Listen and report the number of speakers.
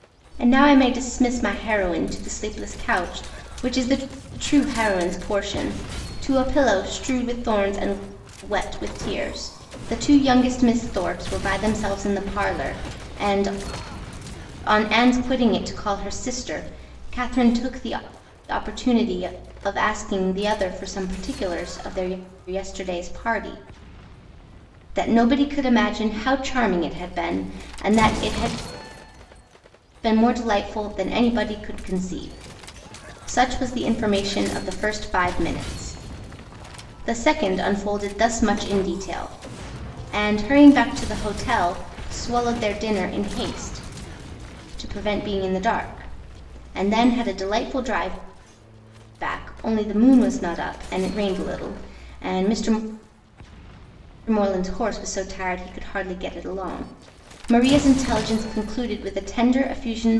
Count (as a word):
one